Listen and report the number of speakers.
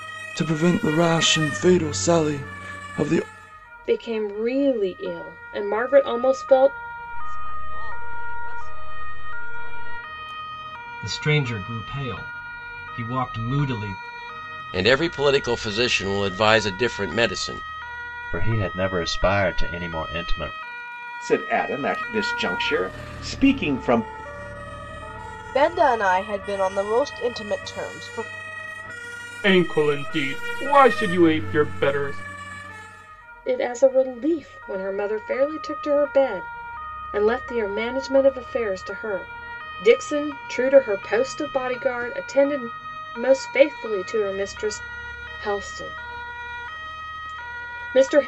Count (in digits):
9